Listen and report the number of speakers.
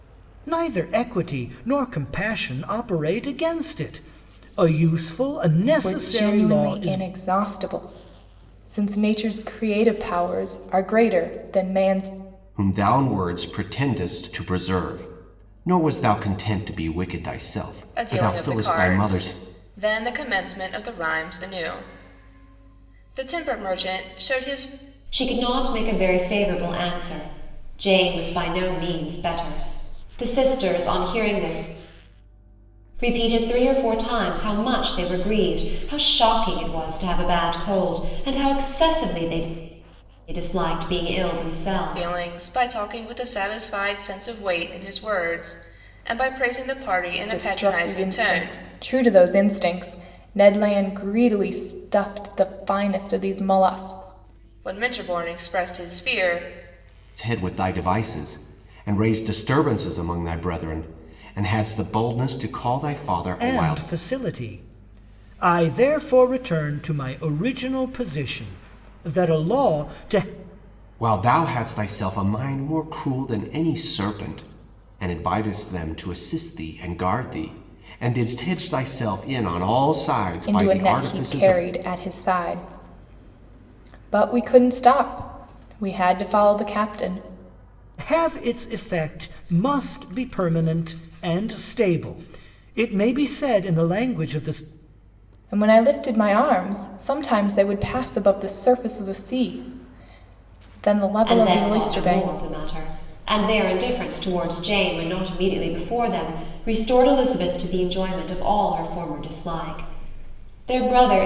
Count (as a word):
five